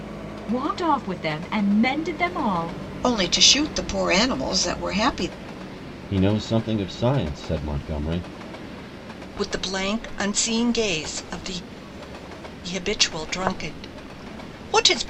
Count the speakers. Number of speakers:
4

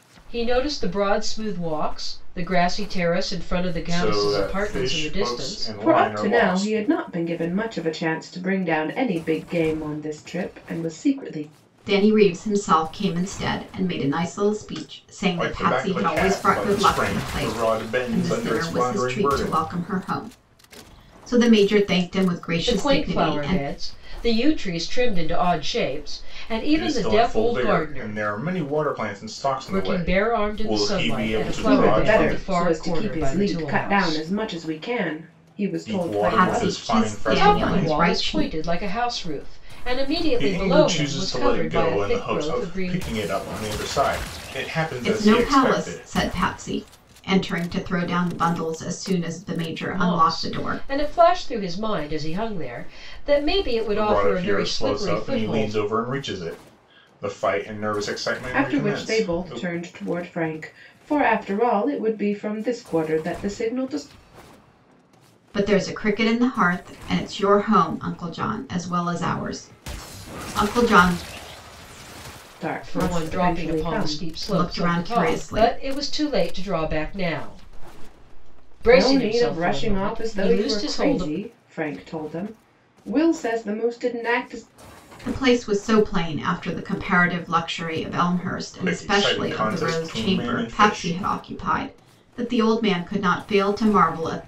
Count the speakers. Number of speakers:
4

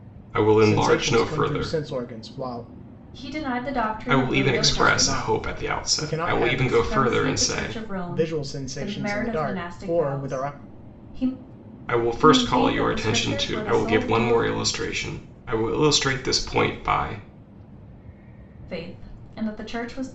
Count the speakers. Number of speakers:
3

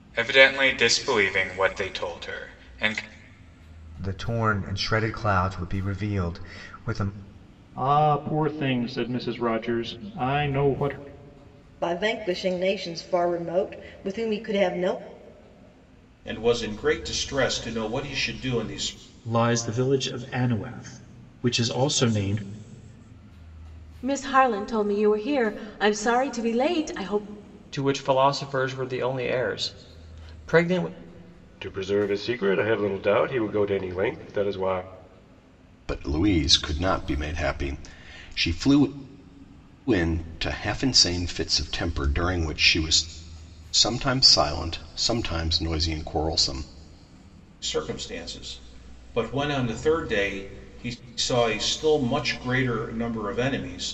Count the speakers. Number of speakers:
10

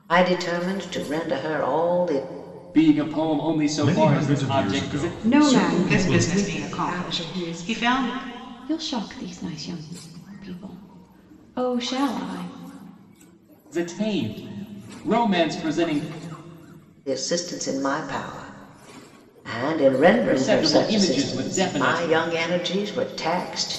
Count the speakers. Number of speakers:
6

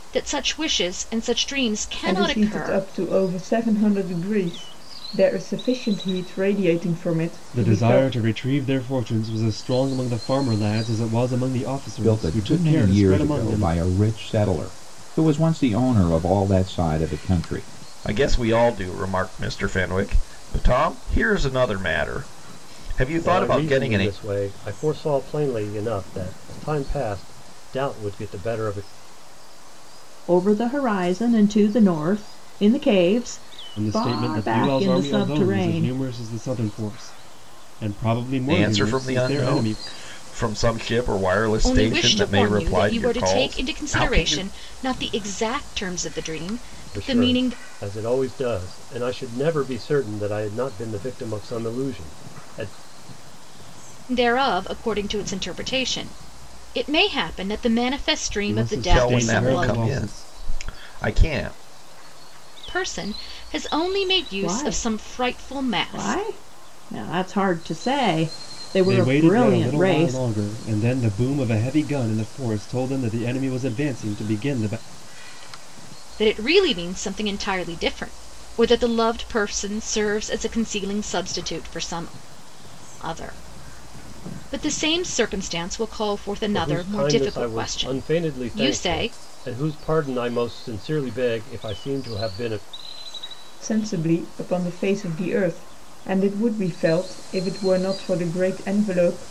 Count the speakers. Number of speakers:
7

